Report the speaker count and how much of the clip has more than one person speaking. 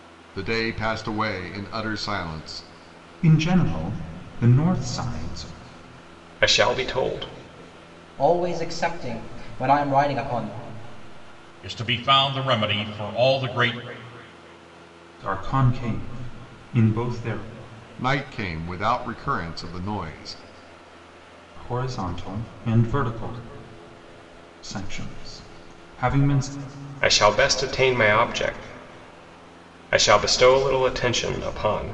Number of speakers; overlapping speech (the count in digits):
5, no overlap